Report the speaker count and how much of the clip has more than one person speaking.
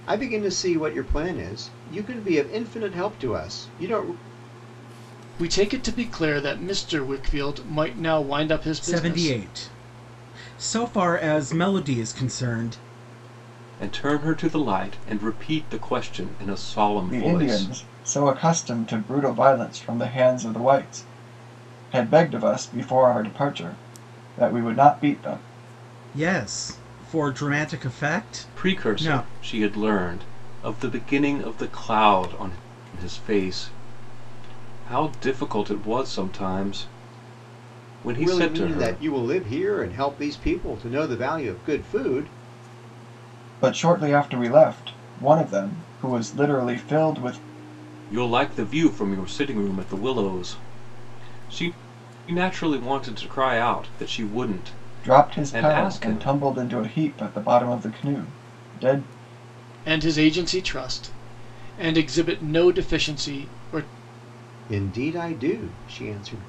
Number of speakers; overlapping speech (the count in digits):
5, about 6%